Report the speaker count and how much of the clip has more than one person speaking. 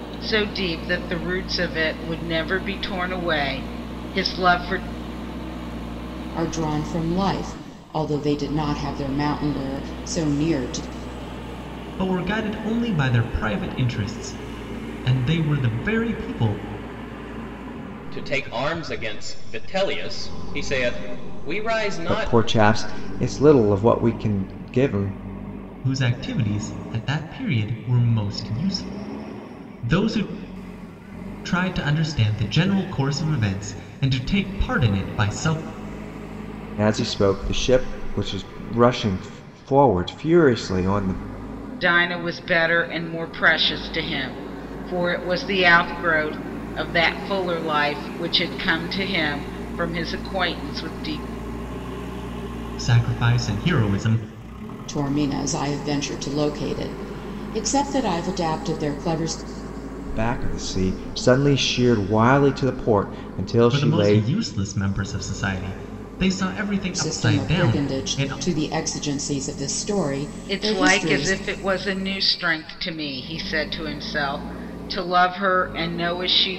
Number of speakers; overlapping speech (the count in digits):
5, about 4%